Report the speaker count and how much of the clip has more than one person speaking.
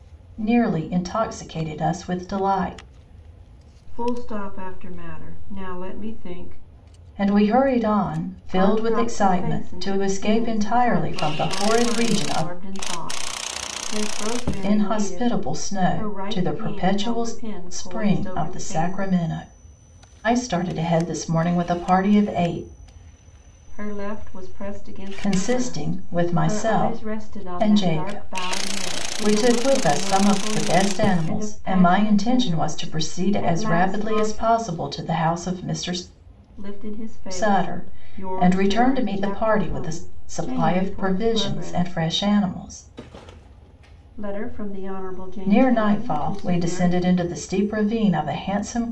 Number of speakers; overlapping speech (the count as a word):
two, about 47%